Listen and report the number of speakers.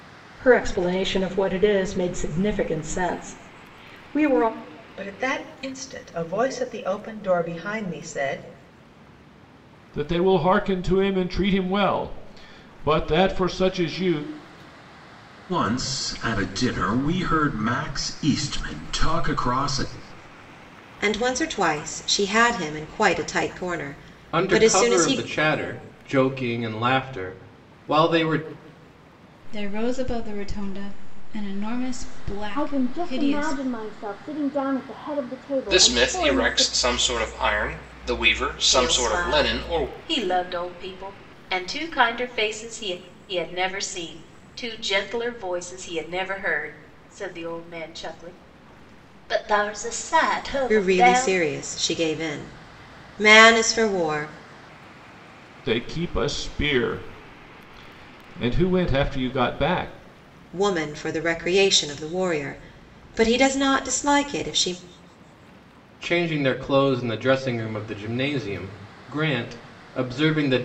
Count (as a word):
ten